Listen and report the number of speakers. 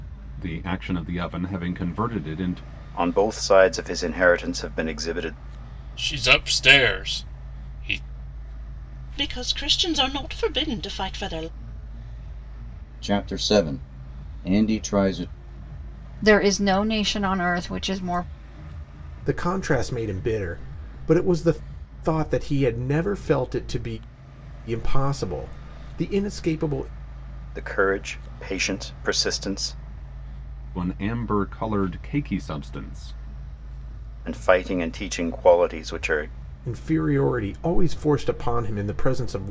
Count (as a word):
seven